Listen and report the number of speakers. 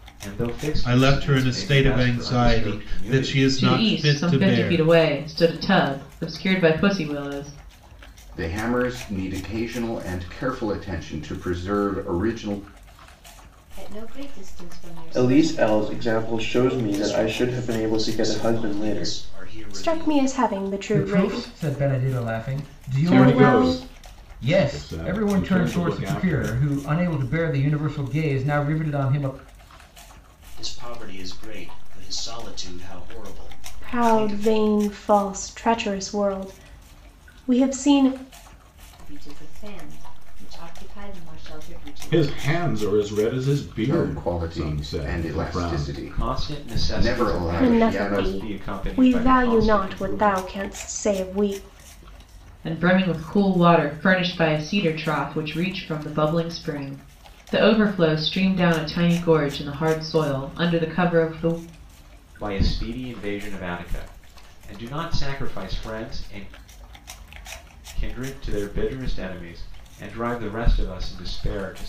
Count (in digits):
10